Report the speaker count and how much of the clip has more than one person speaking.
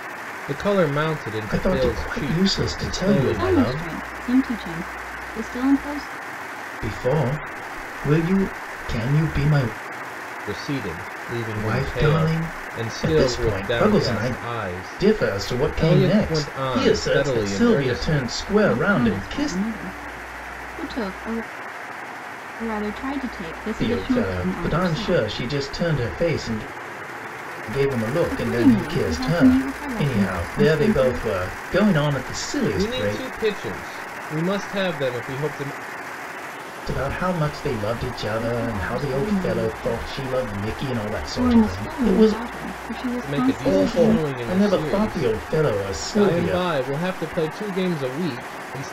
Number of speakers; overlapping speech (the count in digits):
3, about 41%